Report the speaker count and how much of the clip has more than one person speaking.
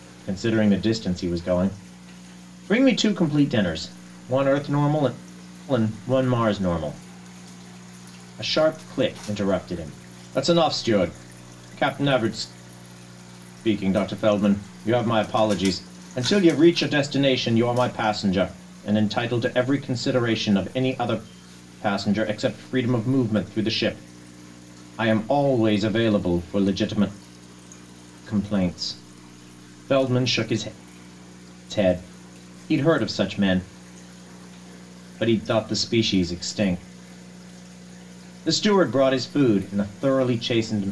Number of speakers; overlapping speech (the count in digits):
1, no overlap